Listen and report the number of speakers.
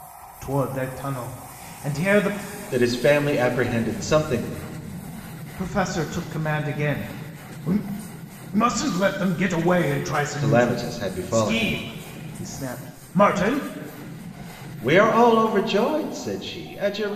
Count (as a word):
two